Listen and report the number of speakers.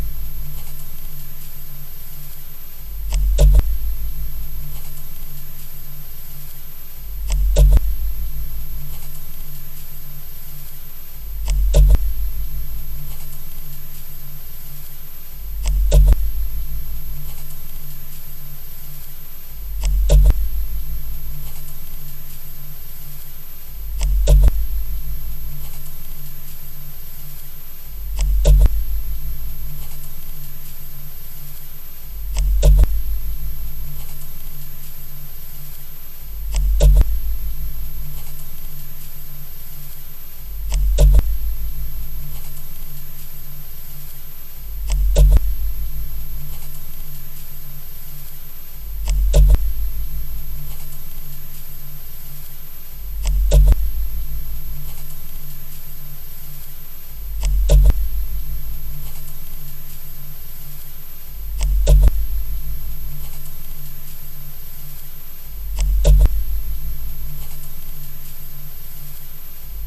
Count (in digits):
0